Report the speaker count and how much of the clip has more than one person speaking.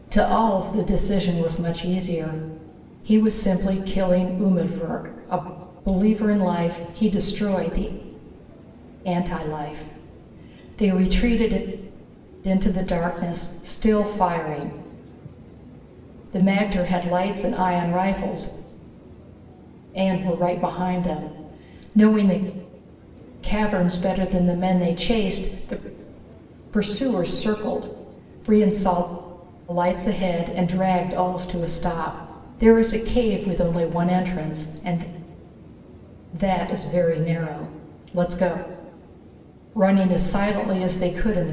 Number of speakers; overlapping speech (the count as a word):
one, no overlap